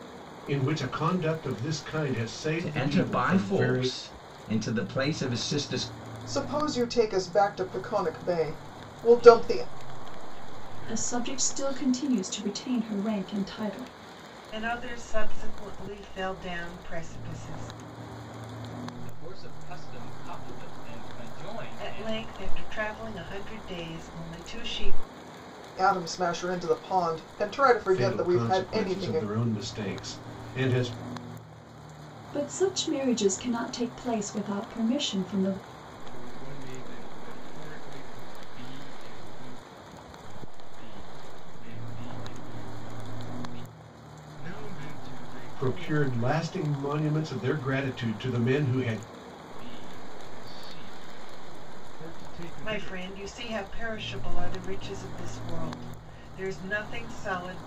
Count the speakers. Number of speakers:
7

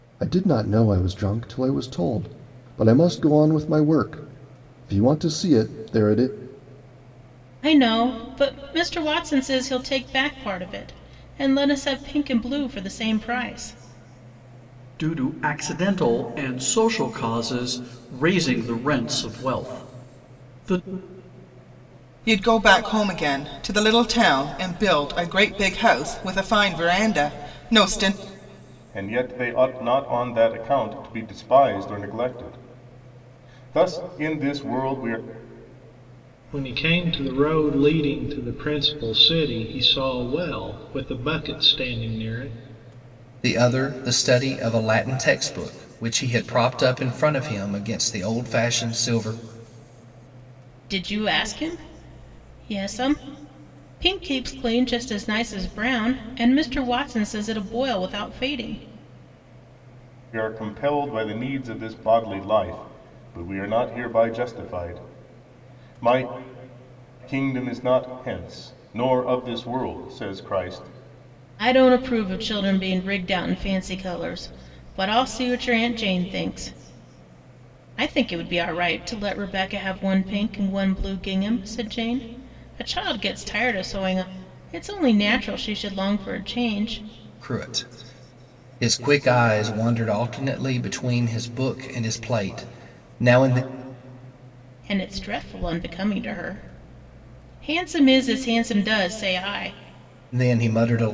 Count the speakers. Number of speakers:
7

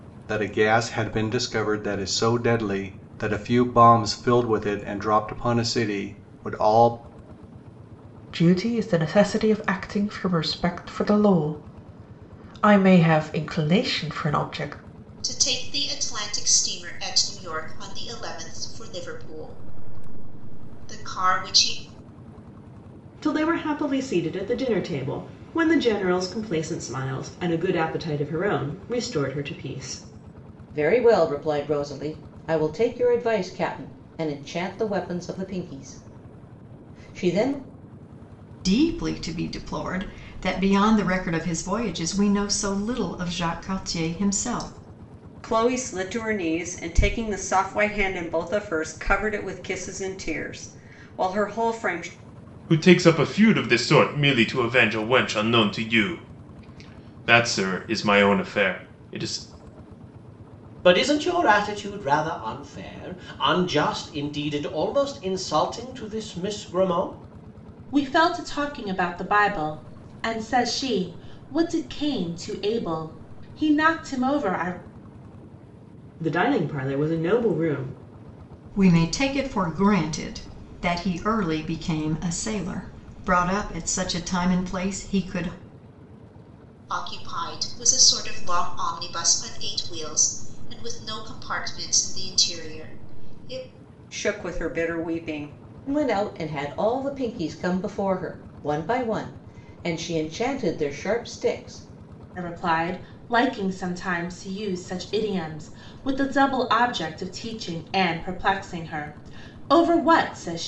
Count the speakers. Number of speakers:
10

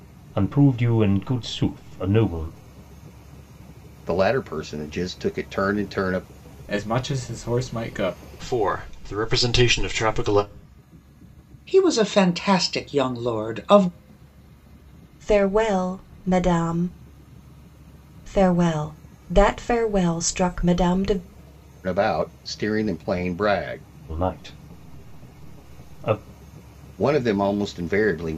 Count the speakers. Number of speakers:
6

